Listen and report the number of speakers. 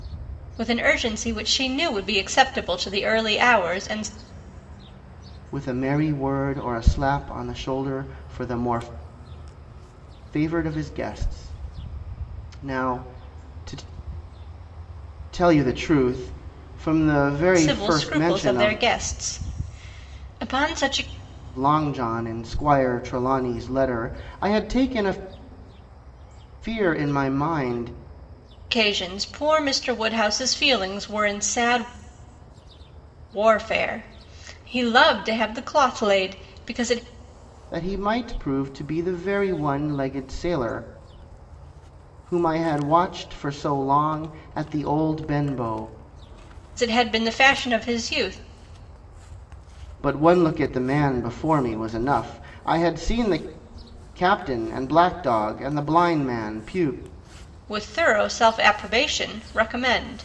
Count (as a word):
two